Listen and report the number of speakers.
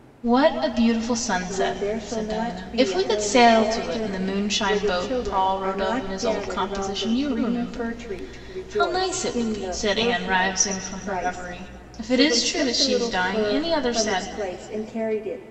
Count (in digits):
2